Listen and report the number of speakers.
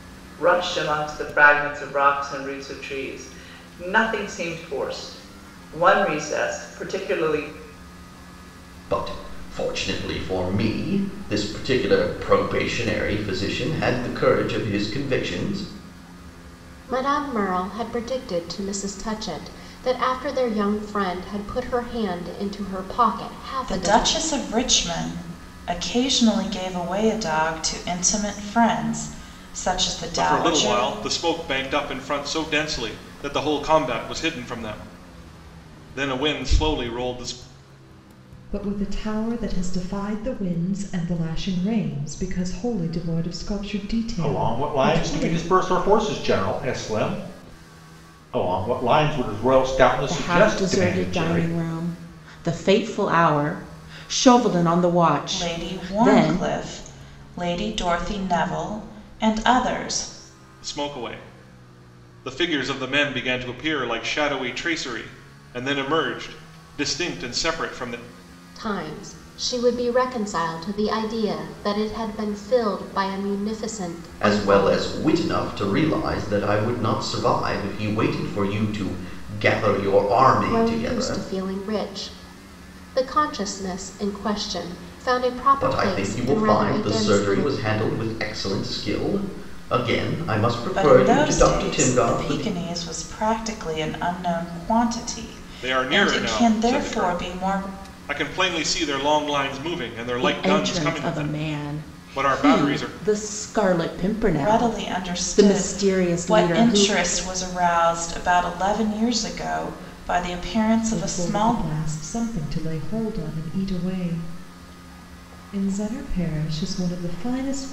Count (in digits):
8